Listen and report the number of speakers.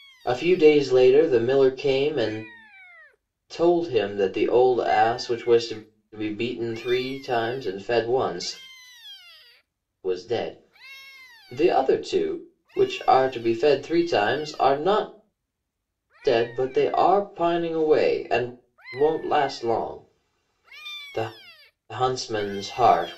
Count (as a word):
one